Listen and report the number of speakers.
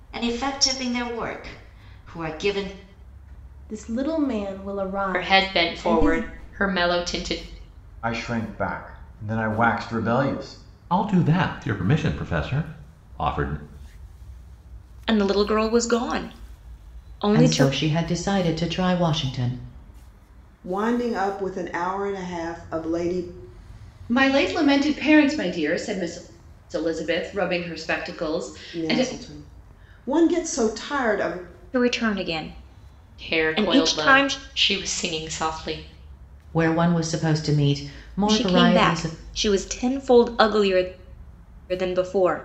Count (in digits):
9